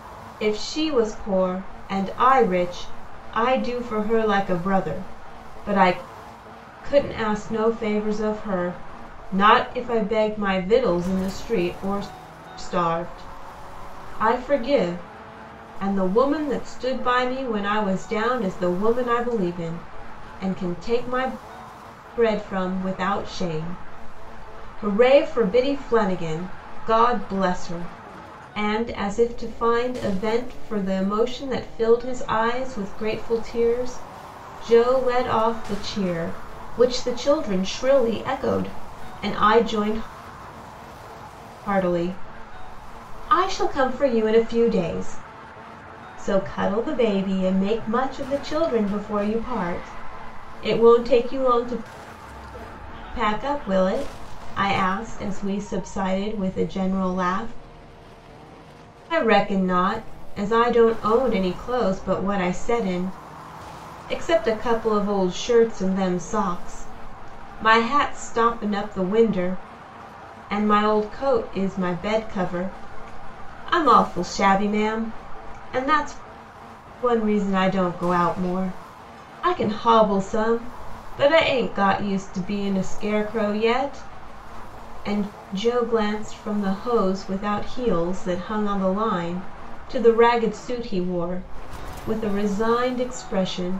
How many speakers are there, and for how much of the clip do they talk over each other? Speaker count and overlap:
1, no overlap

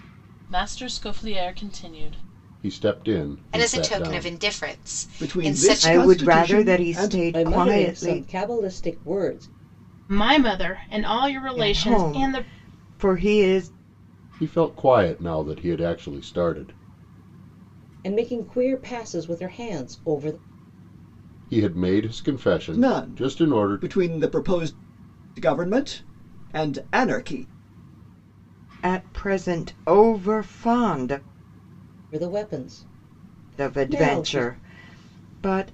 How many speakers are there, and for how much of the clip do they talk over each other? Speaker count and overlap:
7, about 19%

